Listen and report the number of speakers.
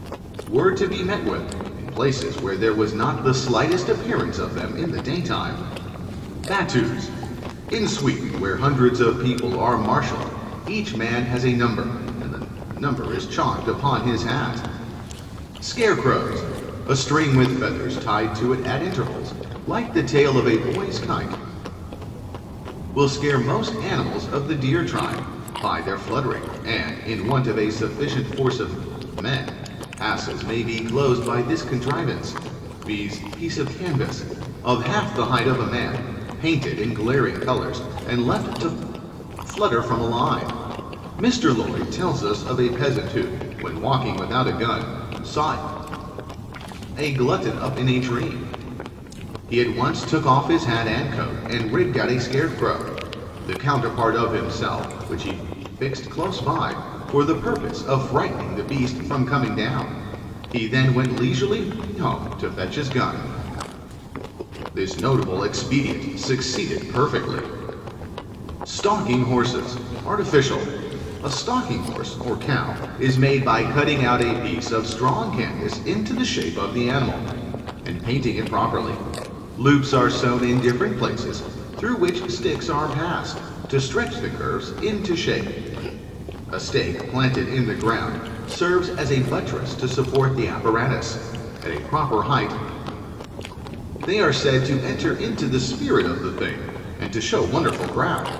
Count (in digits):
1